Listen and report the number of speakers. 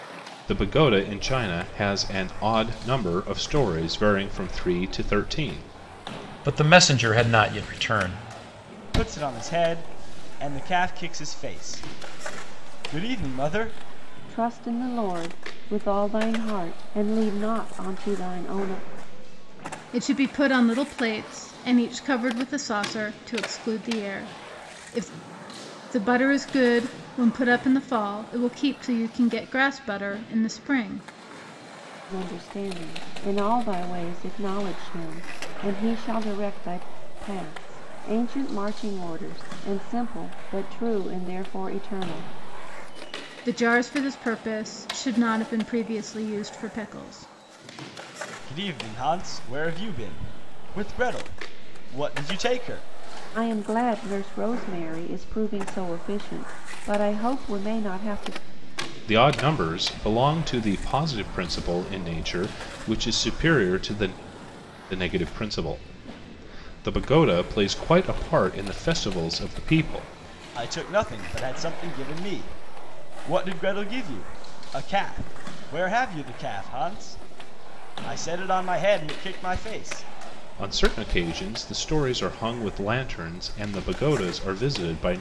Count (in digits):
5